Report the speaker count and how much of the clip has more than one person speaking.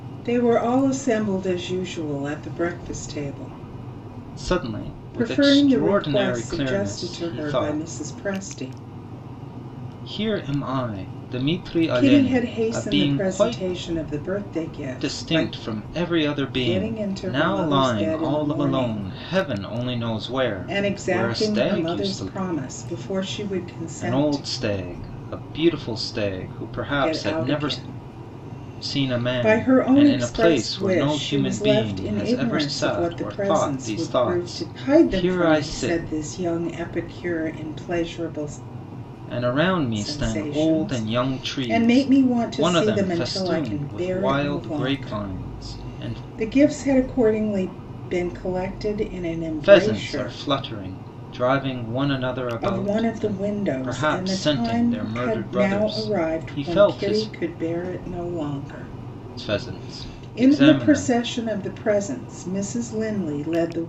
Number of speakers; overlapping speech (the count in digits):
2, about 48%